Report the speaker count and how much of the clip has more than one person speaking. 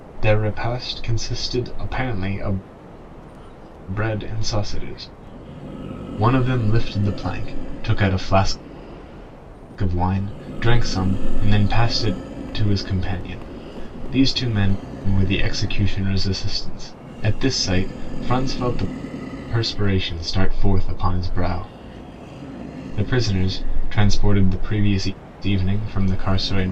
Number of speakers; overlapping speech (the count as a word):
one, no overlap